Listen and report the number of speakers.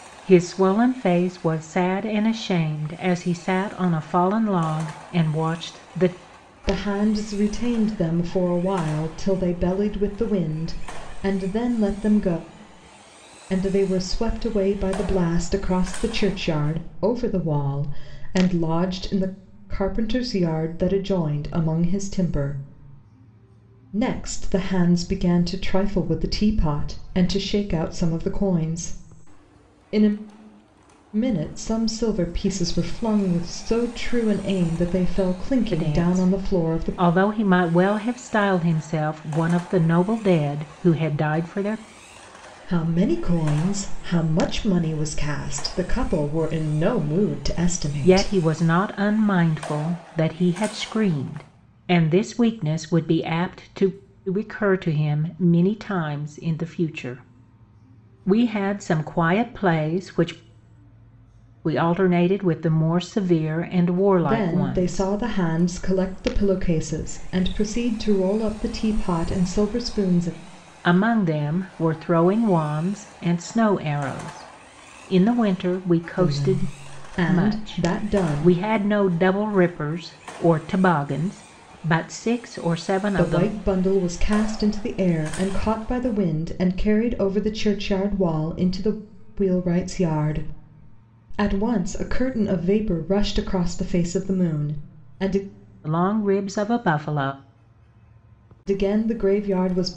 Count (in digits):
2